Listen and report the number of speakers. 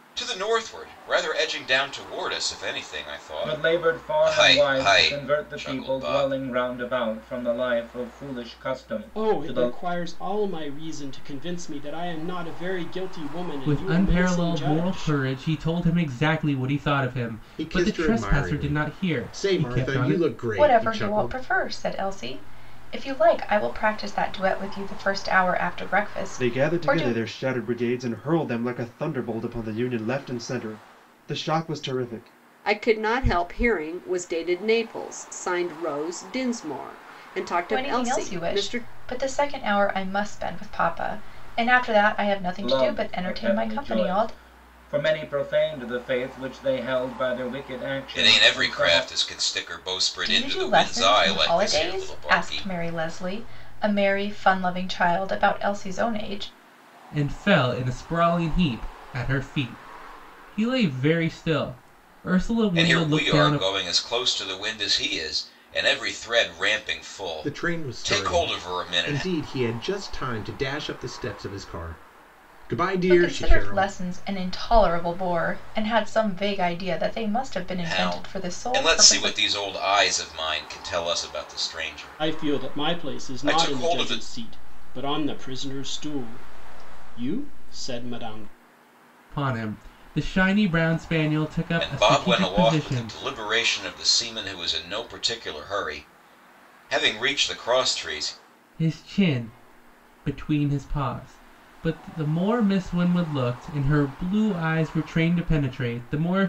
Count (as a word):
eight